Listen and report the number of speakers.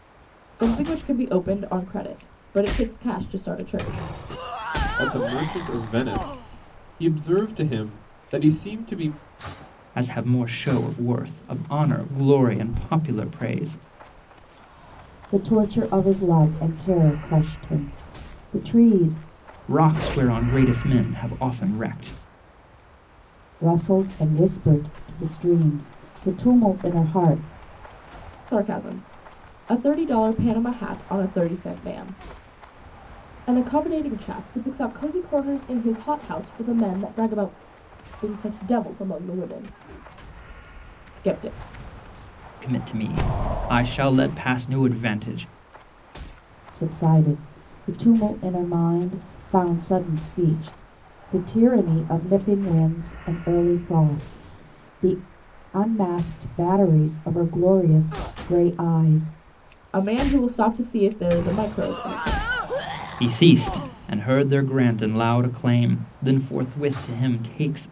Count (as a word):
four